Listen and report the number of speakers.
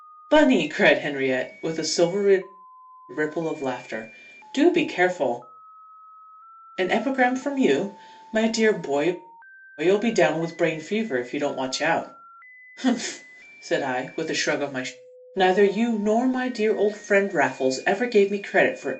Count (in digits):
1